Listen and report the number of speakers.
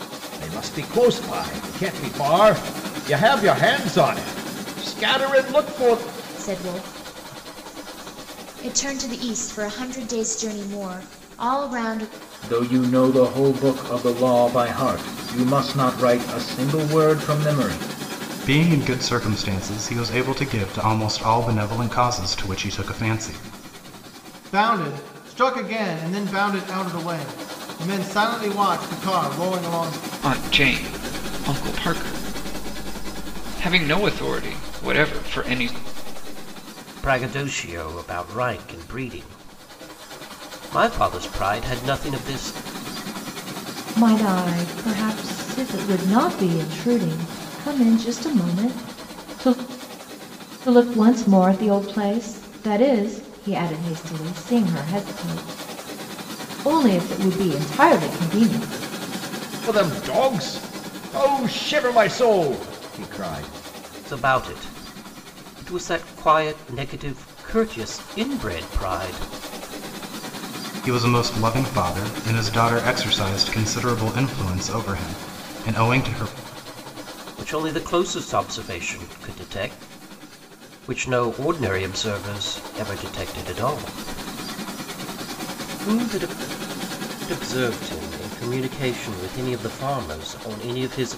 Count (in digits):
8